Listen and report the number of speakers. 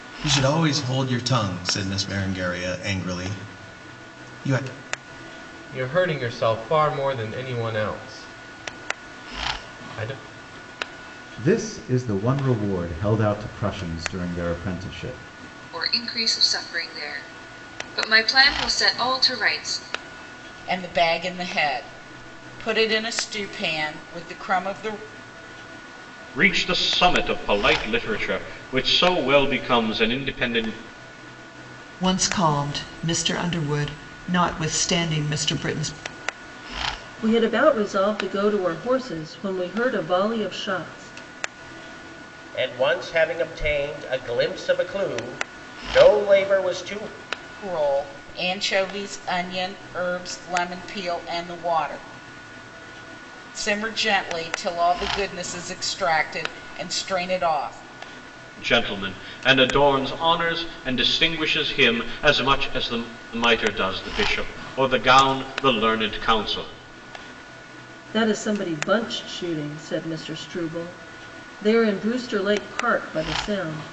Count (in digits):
9